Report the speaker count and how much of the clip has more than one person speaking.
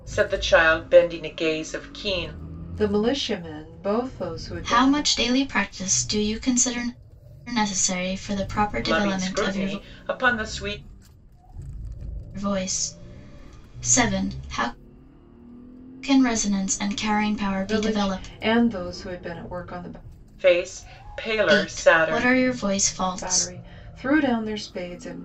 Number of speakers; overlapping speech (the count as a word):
three, about 14%